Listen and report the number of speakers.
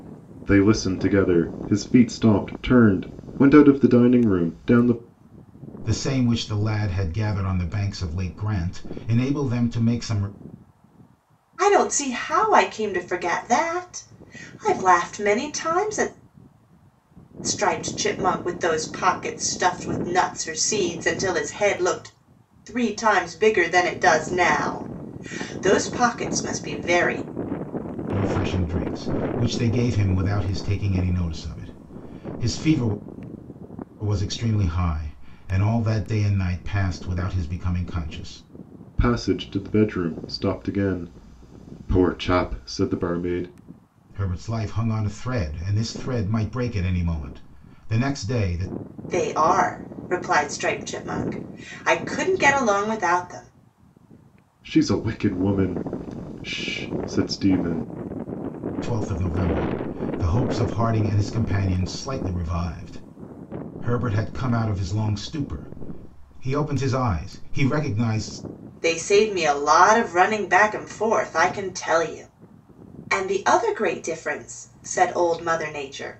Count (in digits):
3